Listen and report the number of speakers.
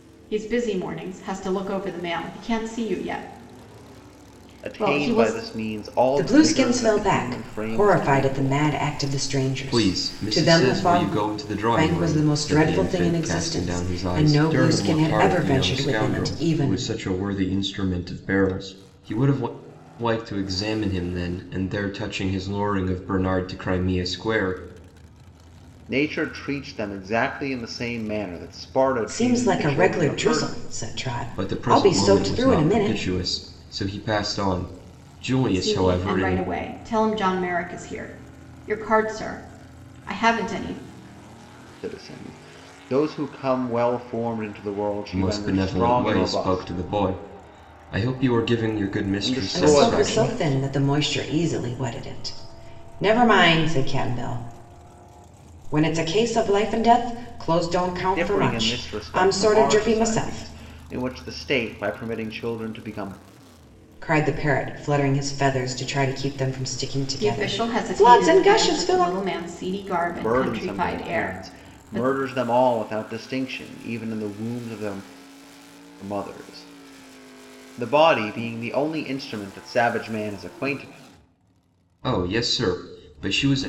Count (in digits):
4